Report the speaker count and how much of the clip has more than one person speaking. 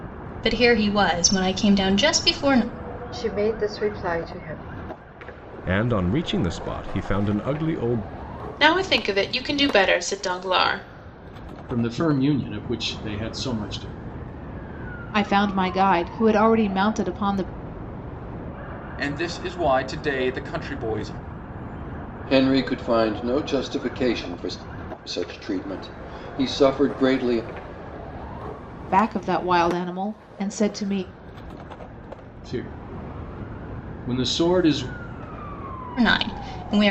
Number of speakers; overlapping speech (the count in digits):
8, no overlap